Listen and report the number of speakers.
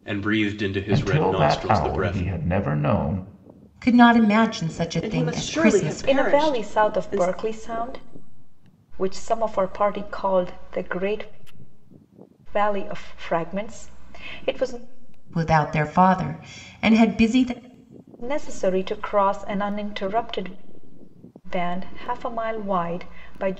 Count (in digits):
5